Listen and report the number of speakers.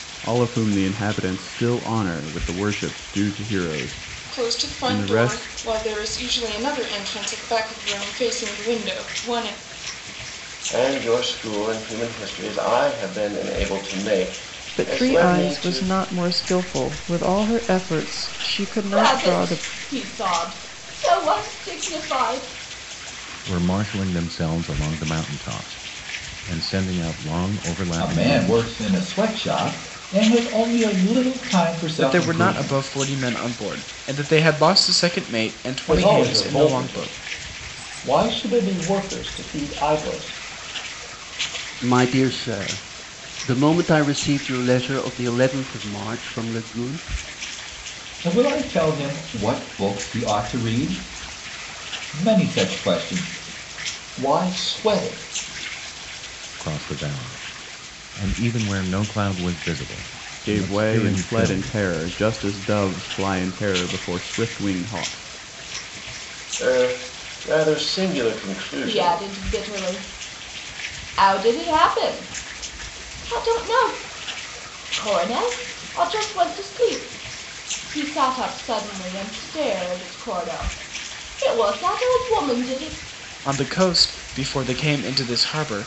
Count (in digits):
10